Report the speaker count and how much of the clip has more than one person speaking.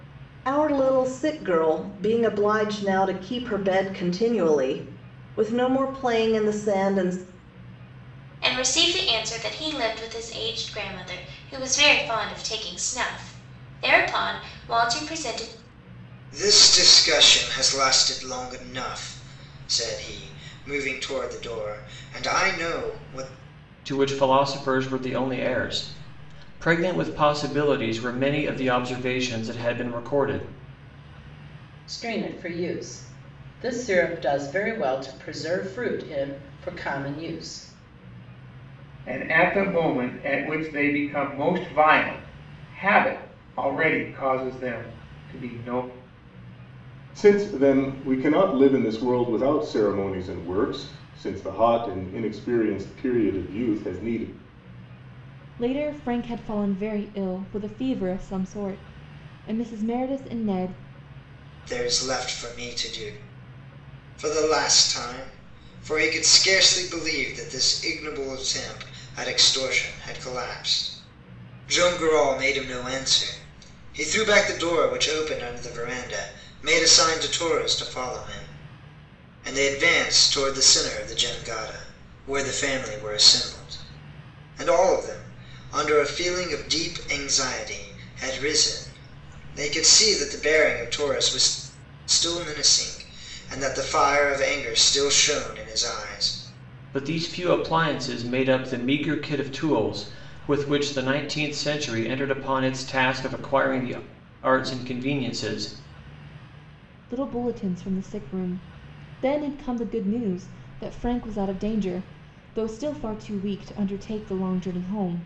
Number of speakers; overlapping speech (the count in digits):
8, no overlap